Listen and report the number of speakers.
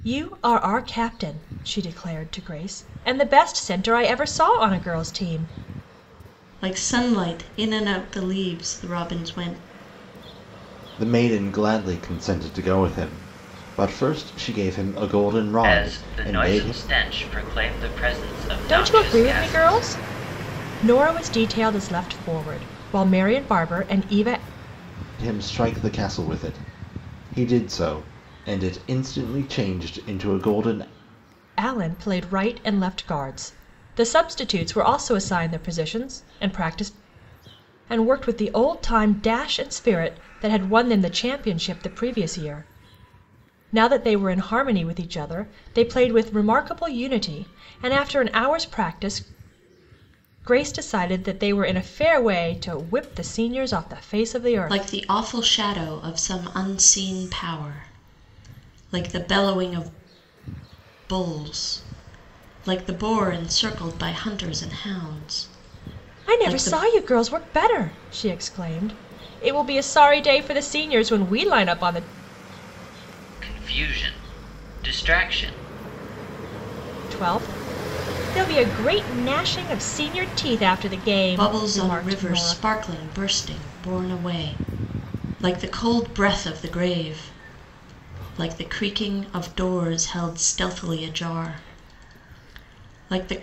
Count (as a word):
four